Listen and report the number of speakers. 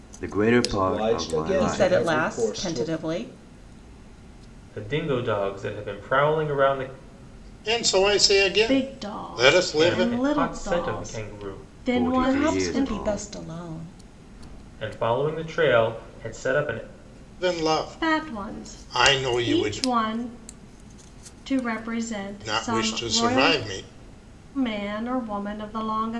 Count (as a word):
six